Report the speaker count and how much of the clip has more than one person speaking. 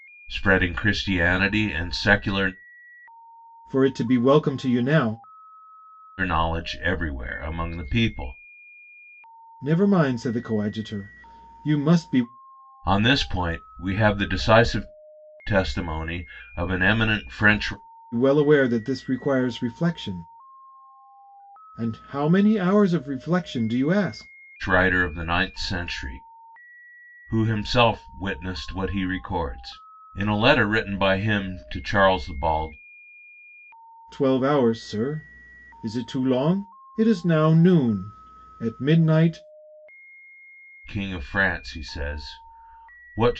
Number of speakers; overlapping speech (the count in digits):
2, no overlap